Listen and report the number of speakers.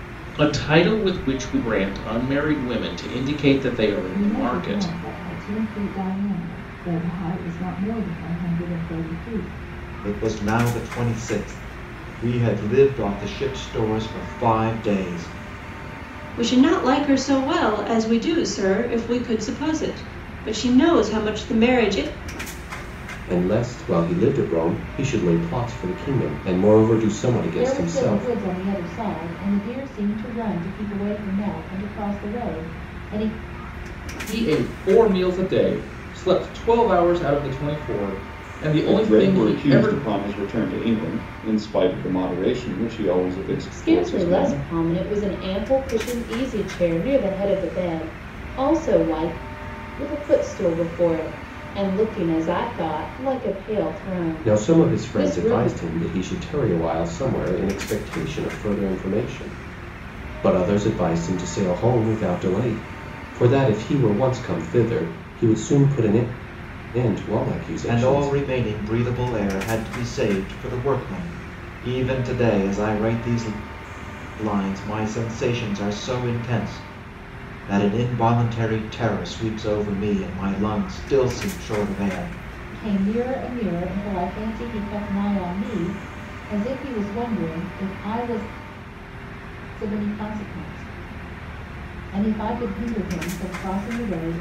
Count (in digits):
9